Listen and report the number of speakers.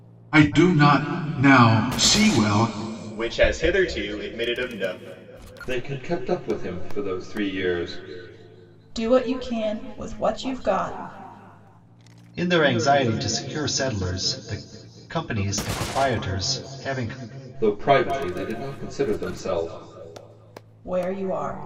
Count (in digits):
5